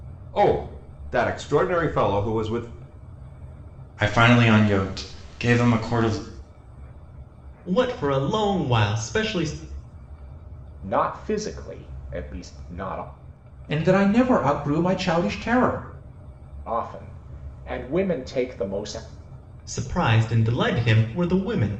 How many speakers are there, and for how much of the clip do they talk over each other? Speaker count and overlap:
five, no overlap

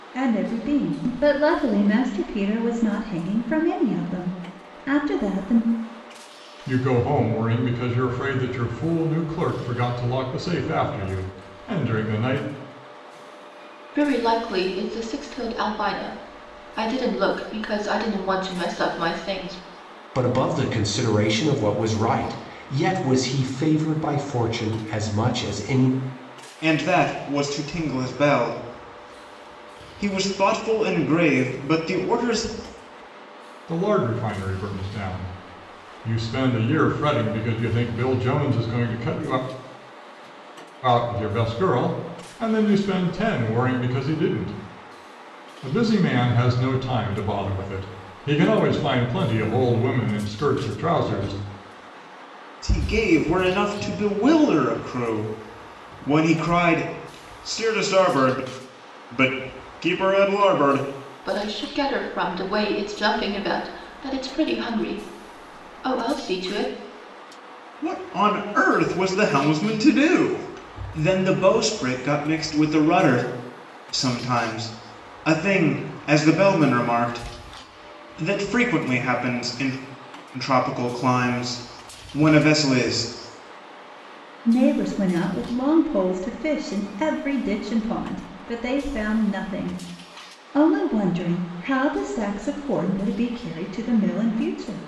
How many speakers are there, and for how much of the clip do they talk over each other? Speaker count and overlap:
five, no overlap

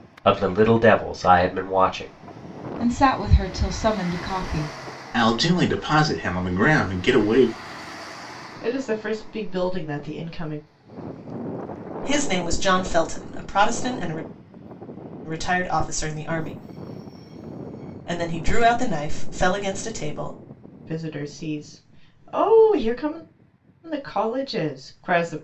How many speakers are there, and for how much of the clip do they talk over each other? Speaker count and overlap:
five, no overlap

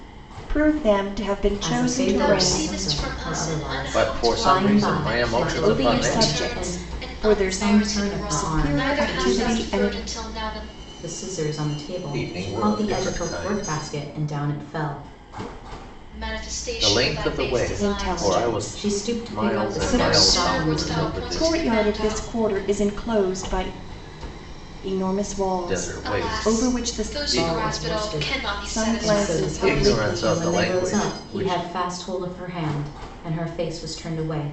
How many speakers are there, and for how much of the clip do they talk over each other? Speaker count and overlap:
four, about 61%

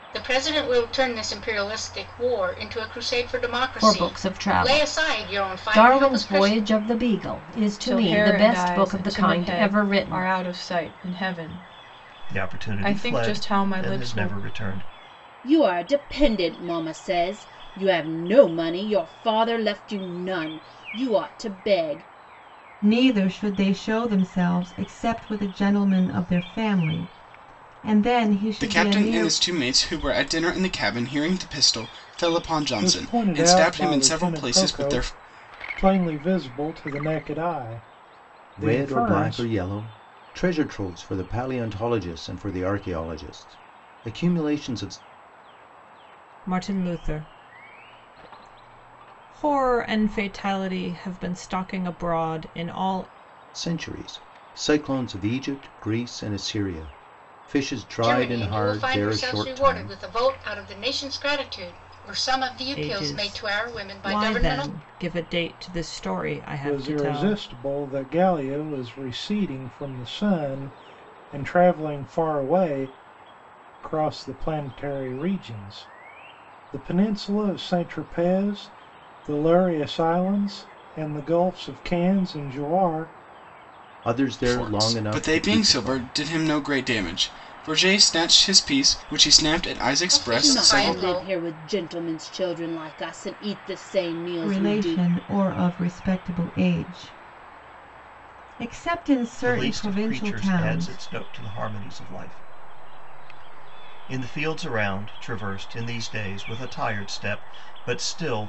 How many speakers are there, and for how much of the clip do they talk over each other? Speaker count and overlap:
ten, about 20%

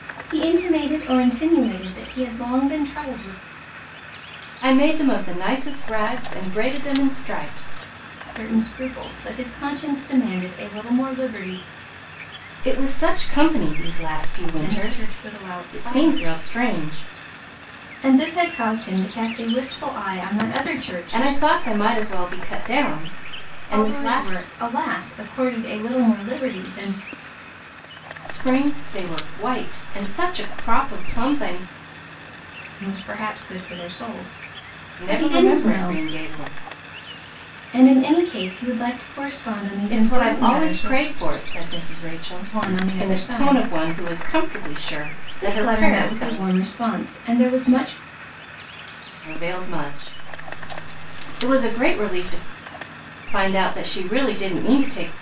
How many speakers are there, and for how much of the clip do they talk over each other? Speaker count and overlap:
two, about 13%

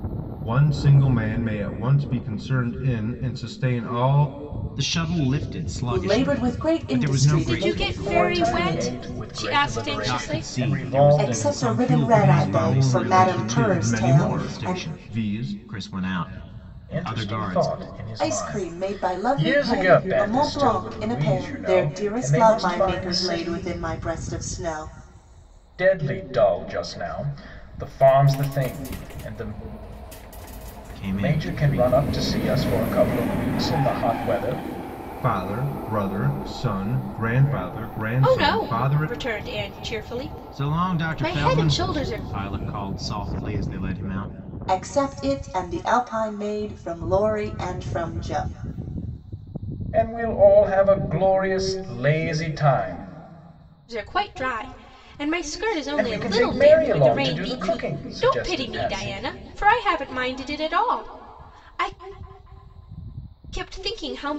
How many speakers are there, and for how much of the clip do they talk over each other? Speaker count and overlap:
five, about 35%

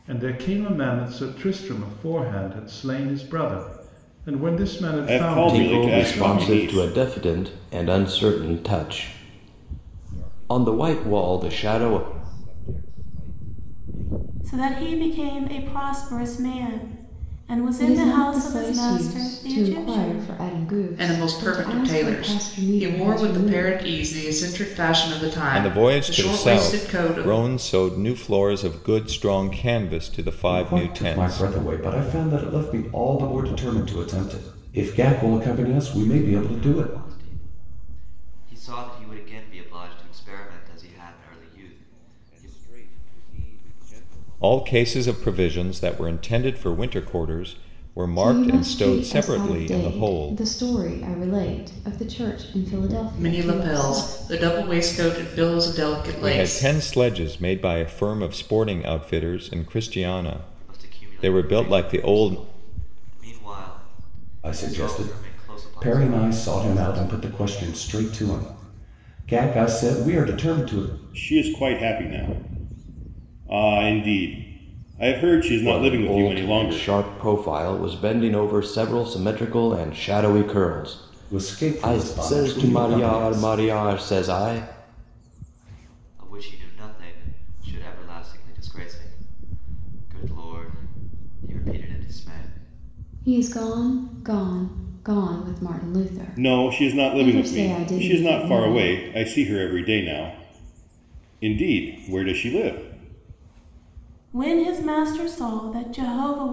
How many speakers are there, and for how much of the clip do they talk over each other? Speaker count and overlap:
ten, about 31%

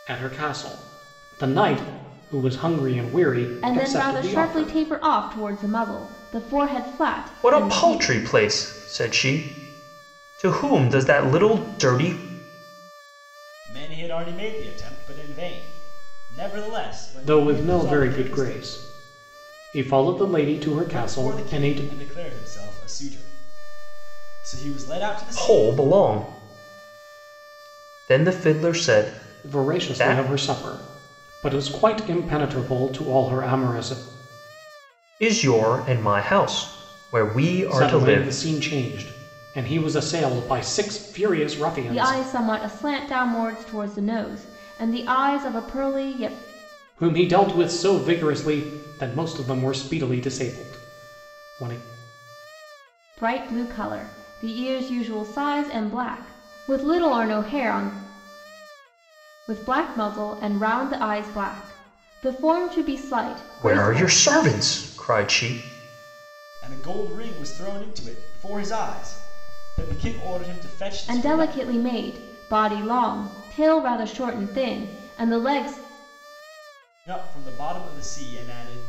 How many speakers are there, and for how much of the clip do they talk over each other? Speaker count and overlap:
four, about 10%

